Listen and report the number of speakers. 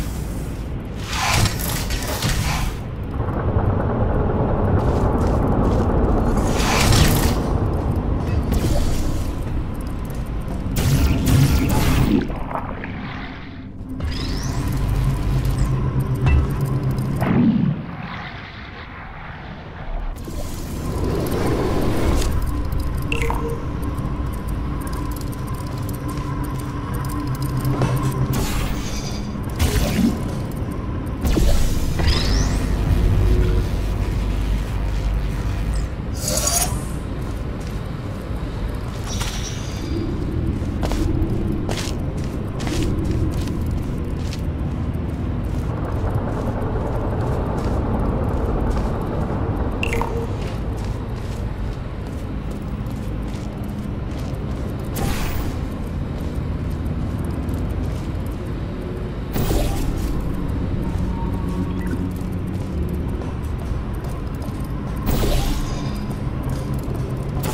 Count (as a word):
zero